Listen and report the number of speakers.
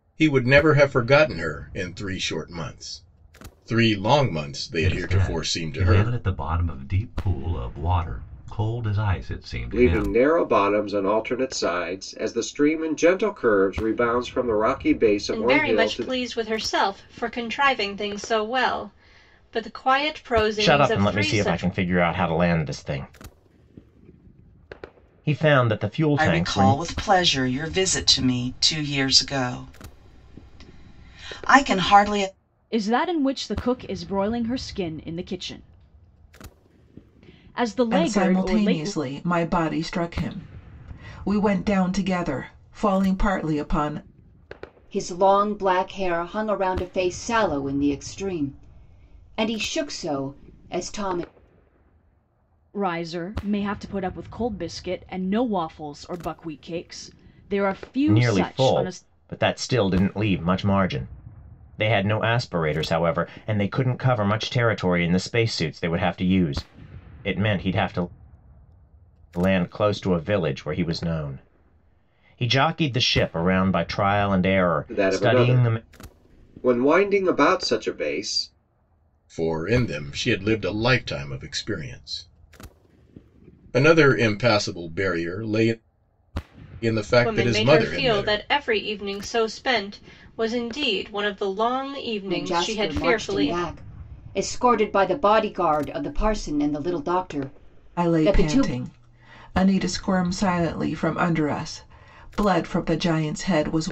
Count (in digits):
9